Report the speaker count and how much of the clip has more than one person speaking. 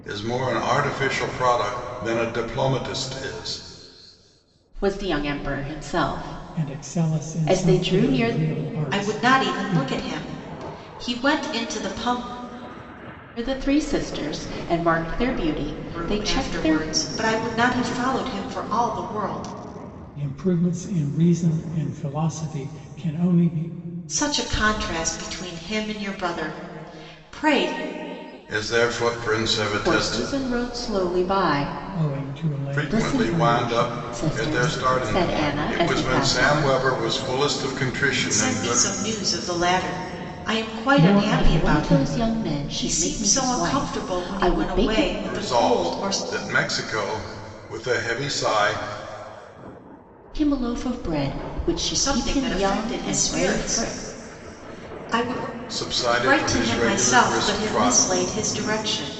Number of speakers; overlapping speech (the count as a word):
four, about 31%